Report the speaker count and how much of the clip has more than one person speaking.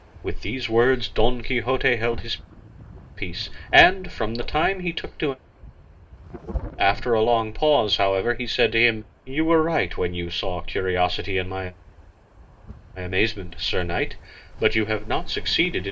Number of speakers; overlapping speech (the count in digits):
1, no overlap